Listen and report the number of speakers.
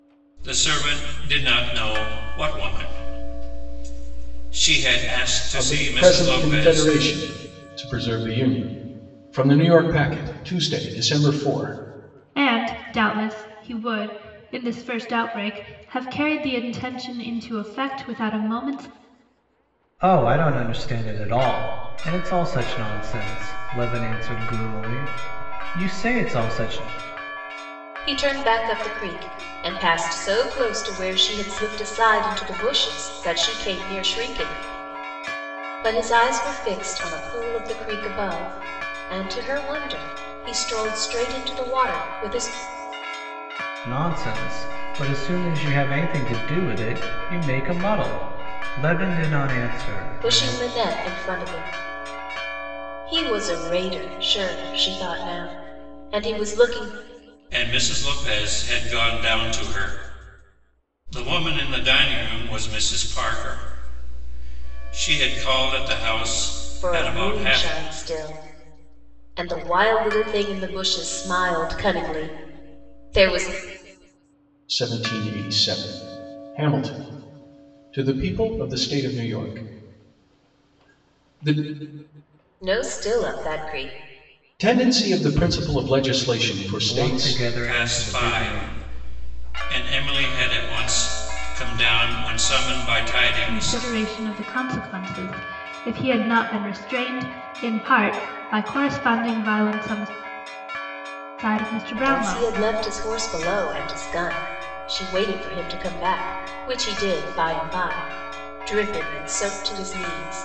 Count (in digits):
5